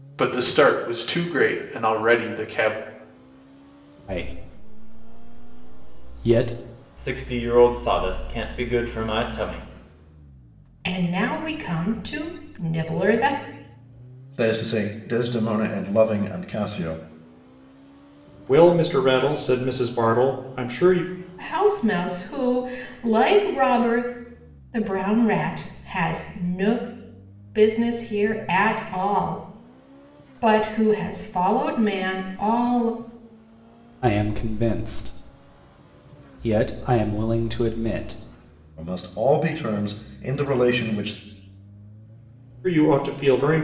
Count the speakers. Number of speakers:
six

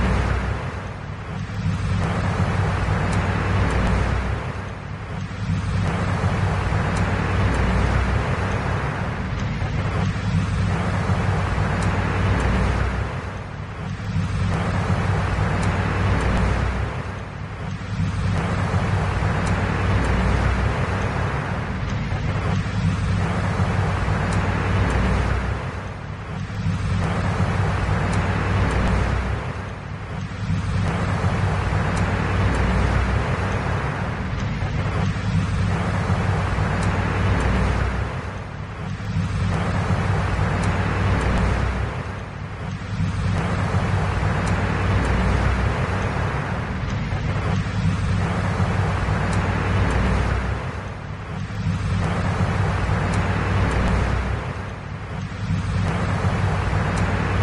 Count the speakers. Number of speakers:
zero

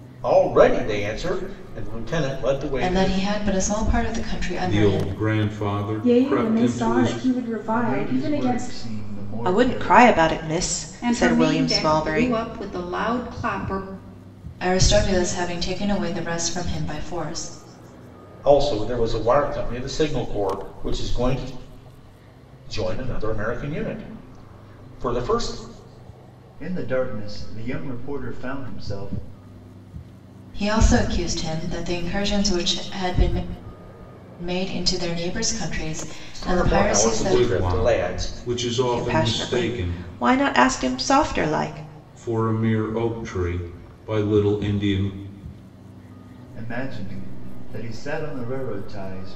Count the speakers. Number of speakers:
seven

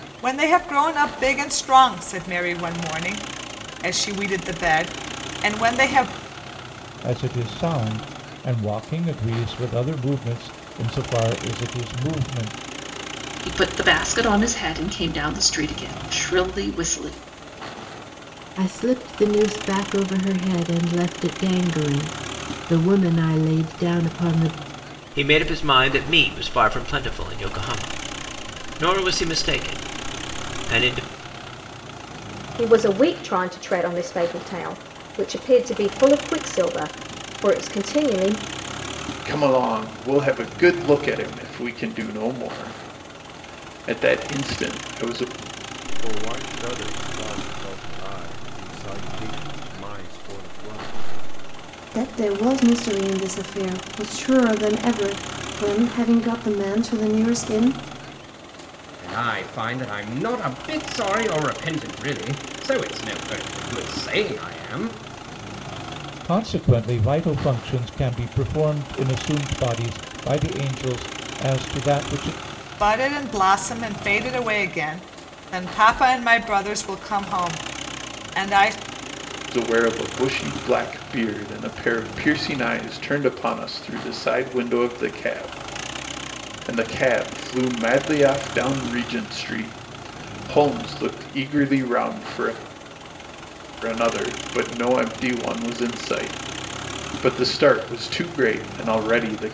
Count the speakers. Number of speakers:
ten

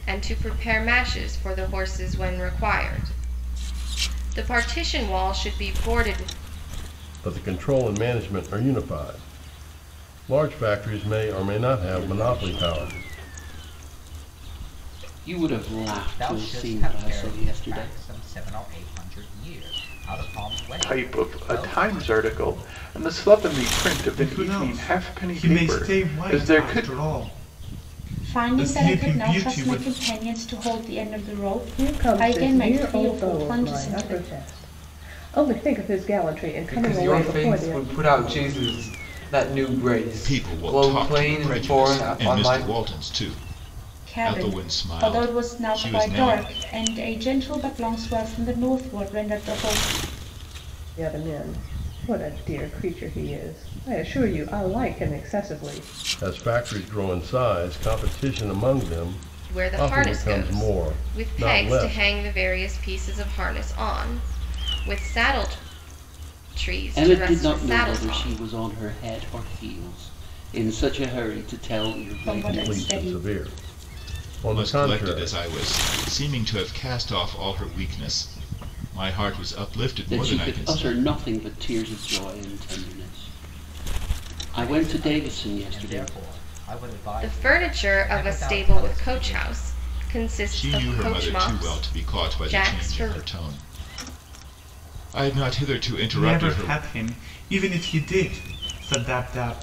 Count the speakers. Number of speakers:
ten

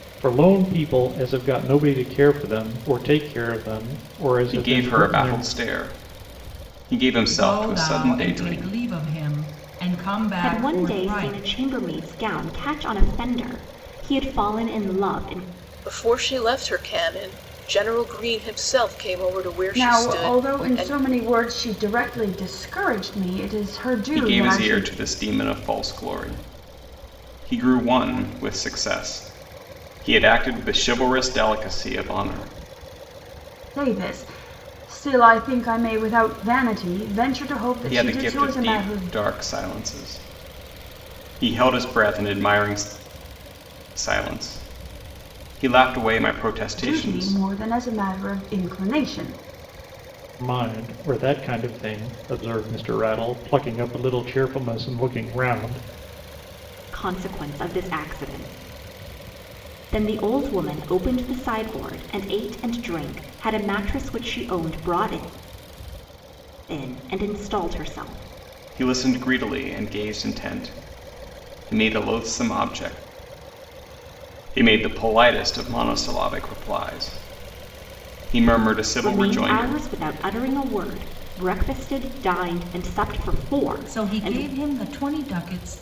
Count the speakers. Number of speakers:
six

